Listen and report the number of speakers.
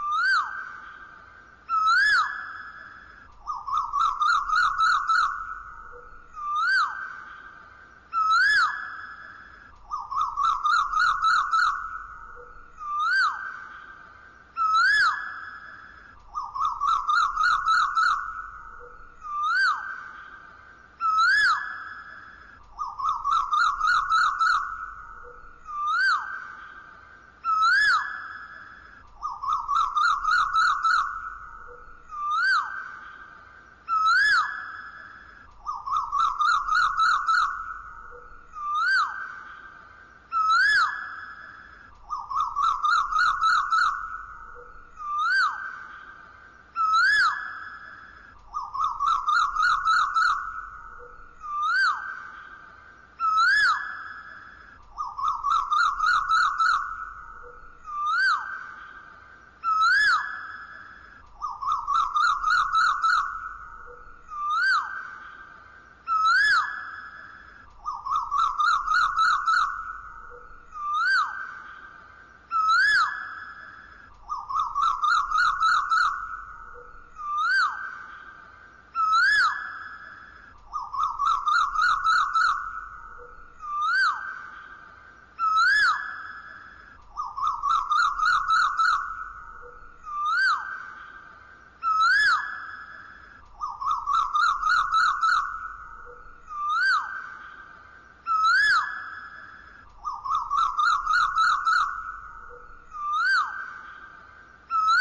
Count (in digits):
0